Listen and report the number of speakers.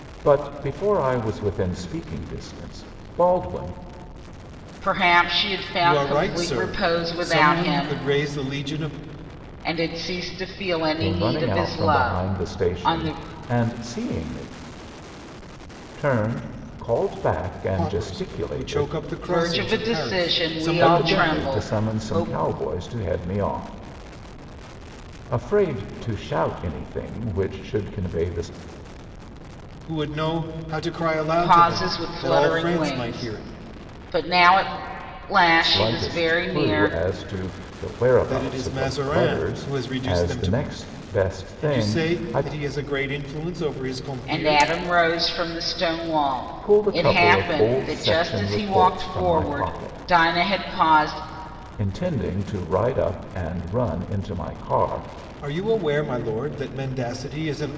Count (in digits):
3